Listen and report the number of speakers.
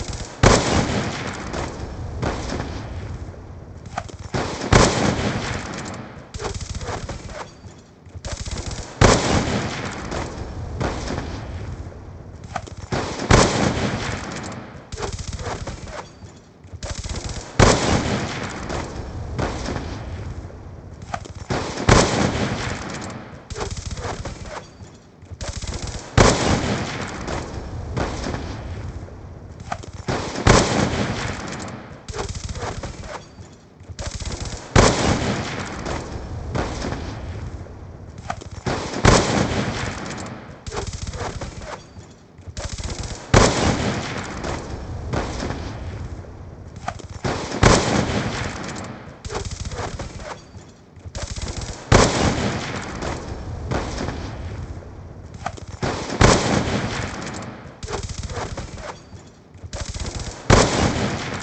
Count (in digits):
0